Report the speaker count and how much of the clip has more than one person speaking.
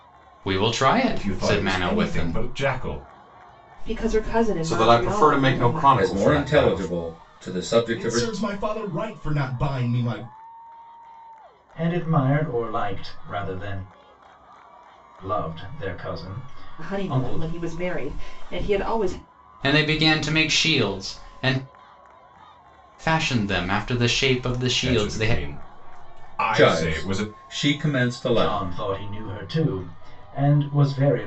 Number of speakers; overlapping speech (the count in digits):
7, about 21%